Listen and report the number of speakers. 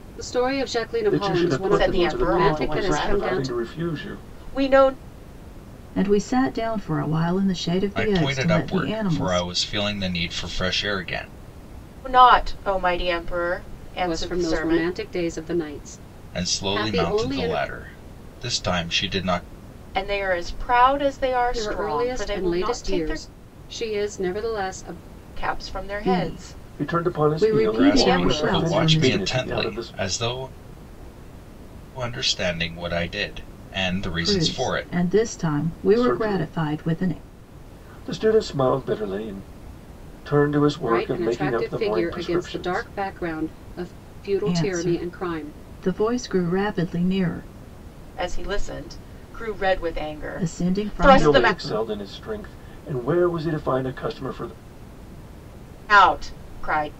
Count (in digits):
5